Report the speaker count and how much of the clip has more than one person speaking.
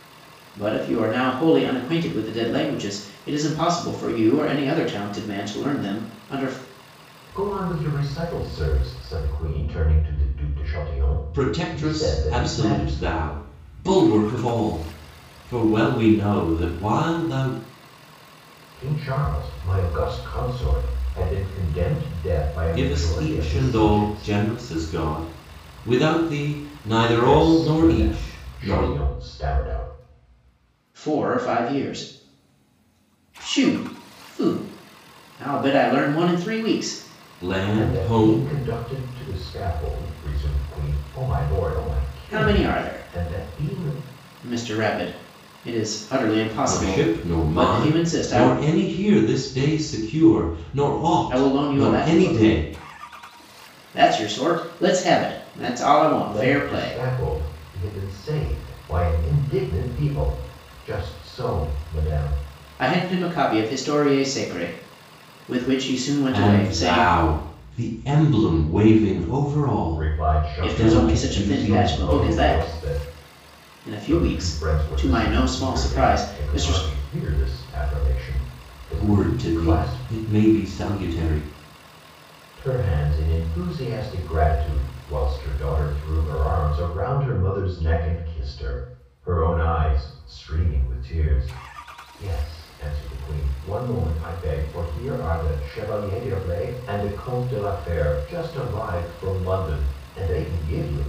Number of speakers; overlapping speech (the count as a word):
three, about 20%